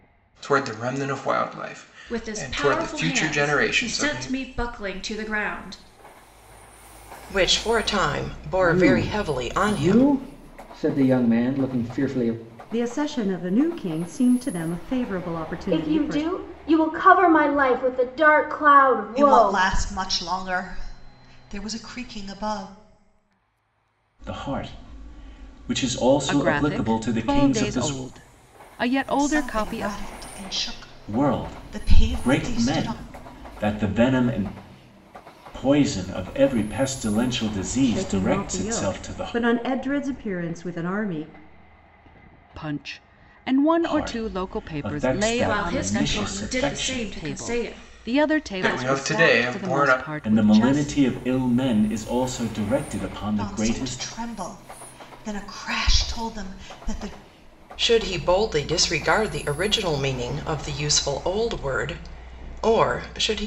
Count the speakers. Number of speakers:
9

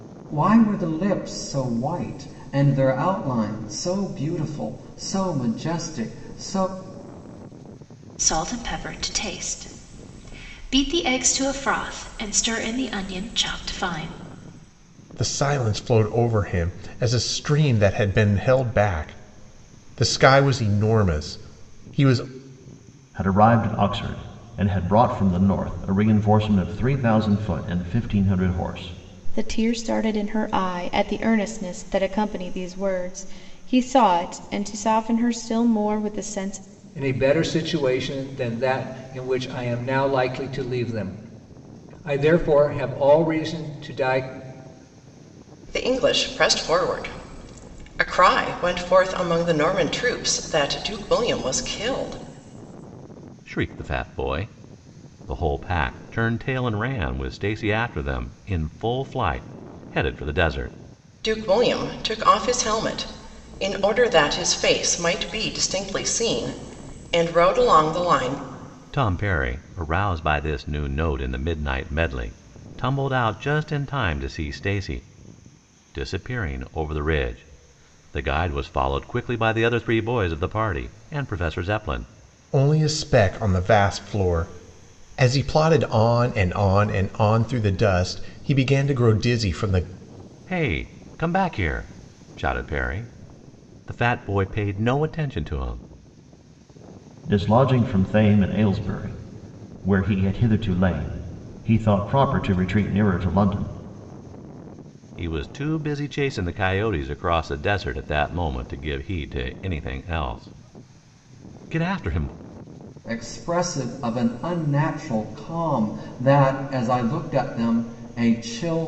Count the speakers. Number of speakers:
8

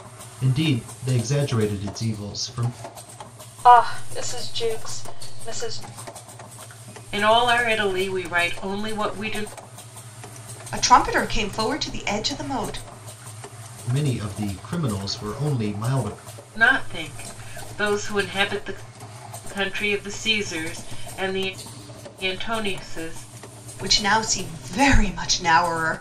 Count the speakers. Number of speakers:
4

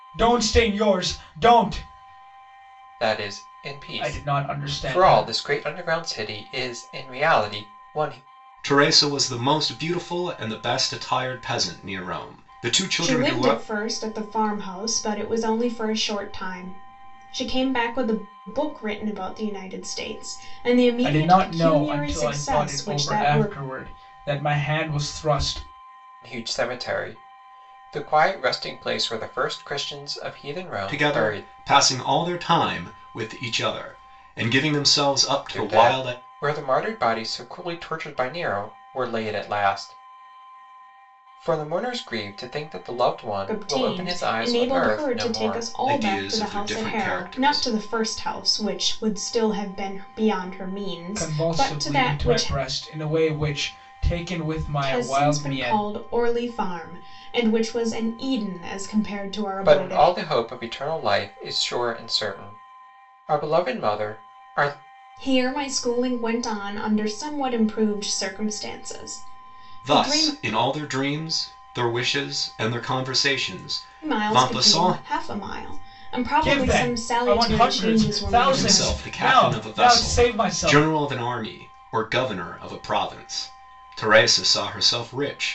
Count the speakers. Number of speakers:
4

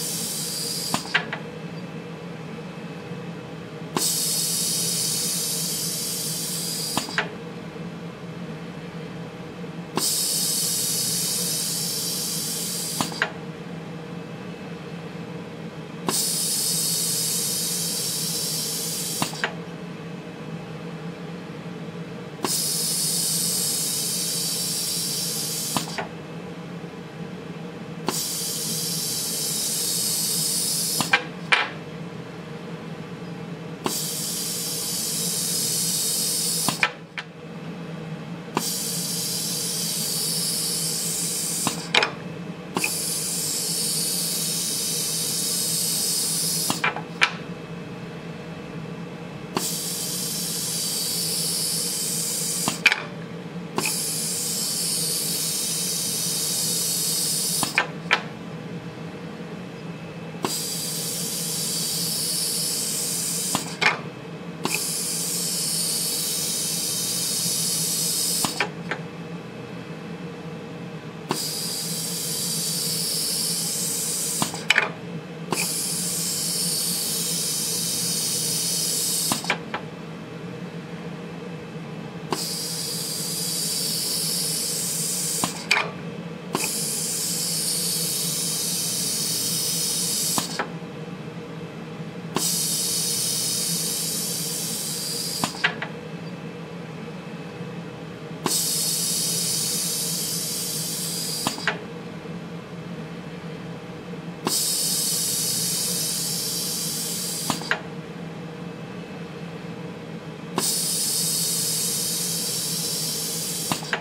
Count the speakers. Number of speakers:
0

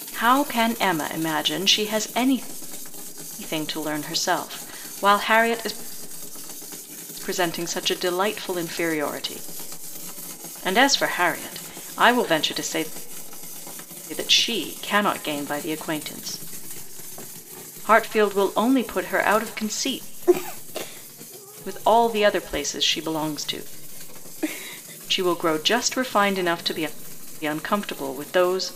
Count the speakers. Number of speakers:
1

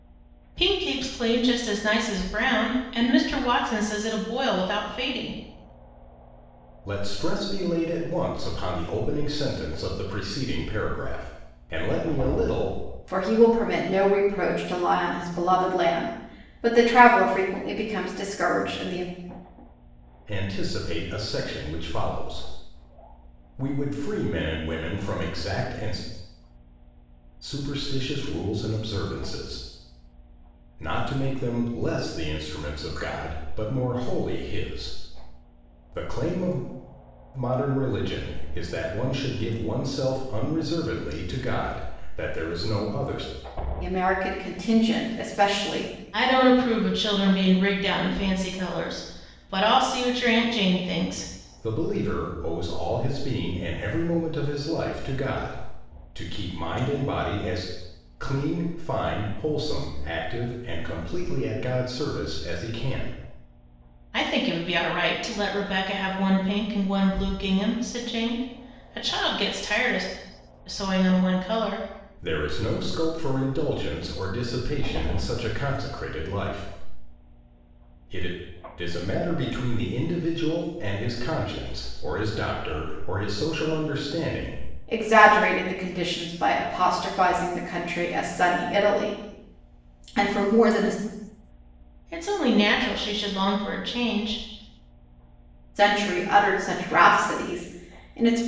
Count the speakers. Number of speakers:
3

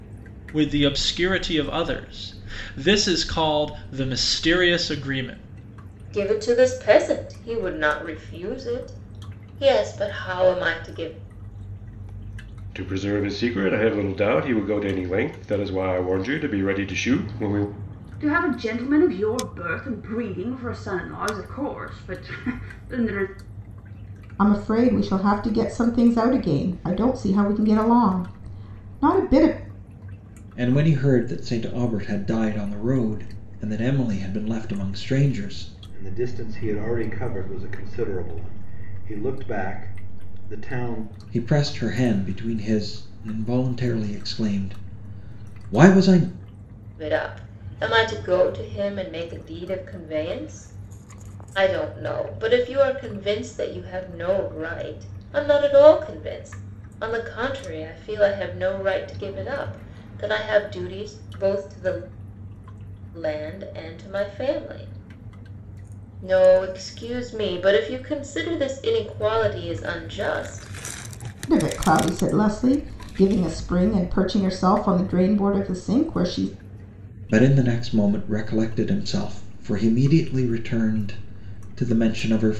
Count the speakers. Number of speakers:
7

